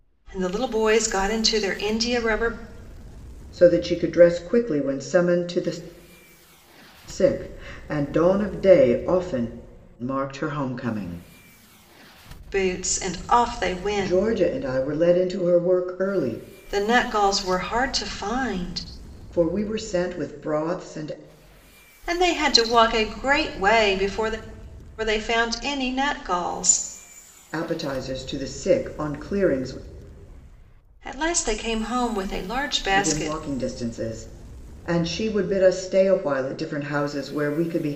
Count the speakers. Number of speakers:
2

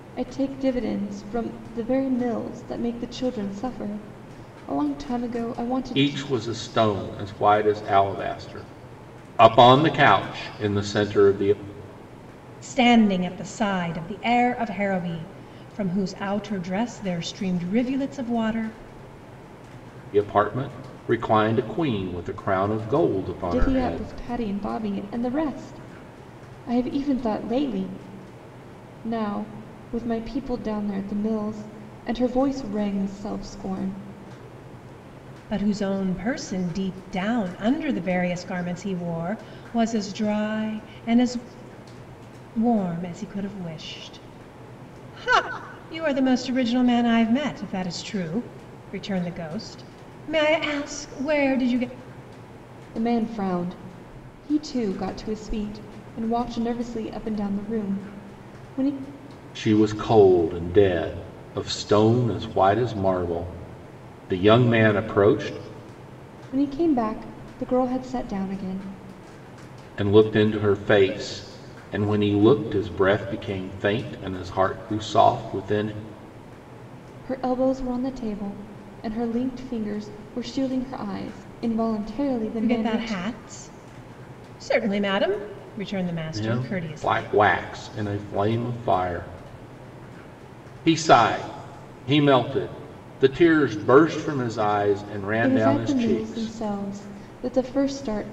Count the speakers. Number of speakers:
3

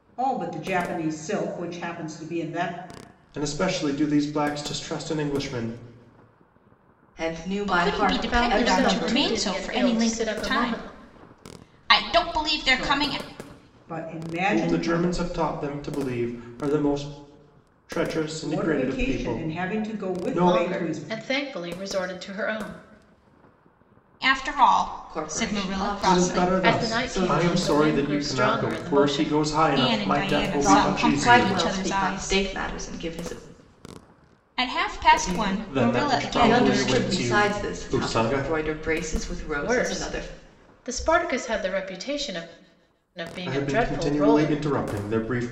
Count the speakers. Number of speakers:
5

